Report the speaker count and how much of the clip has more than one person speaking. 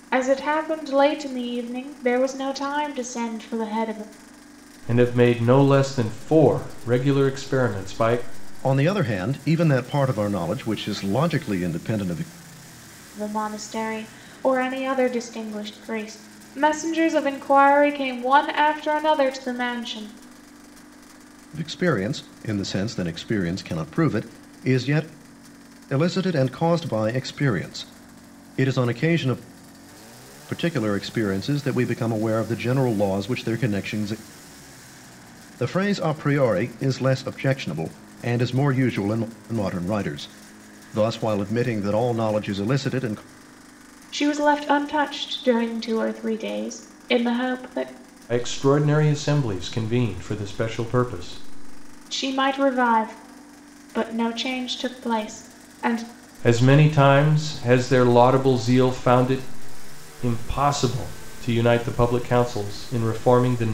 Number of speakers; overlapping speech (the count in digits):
3, no overlap